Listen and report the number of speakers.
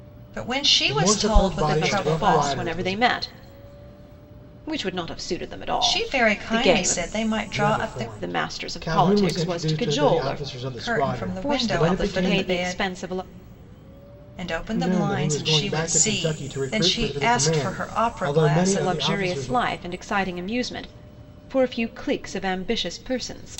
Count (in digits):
3